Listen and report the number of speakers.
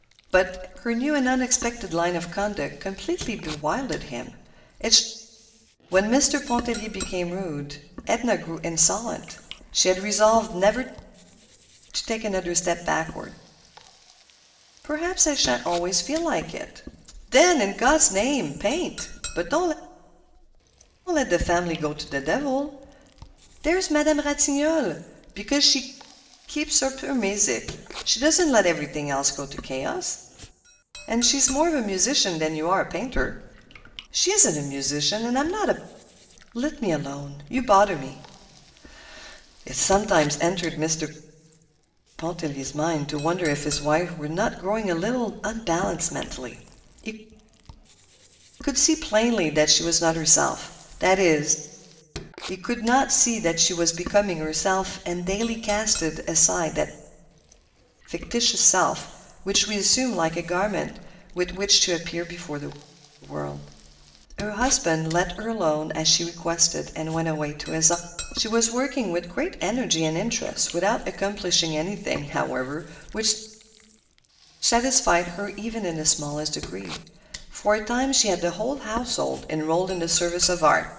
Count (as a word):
one